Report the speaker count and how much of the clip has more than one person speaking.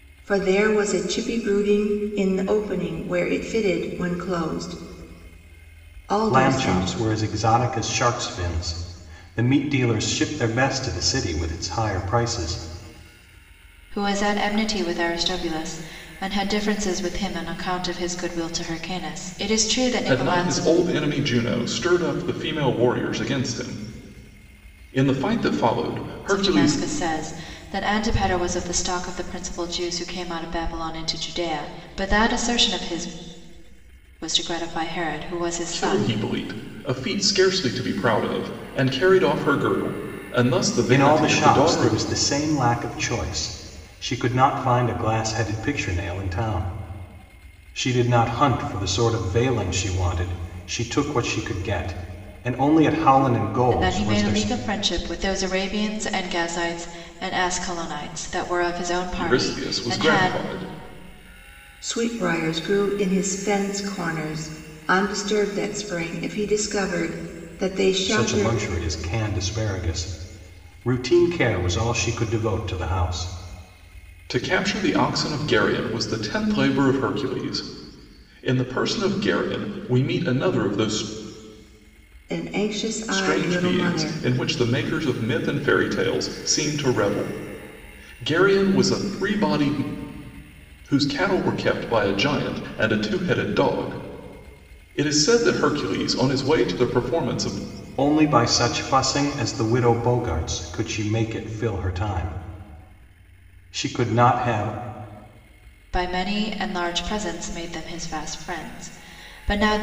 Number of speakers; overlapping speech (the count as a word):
four, about 7%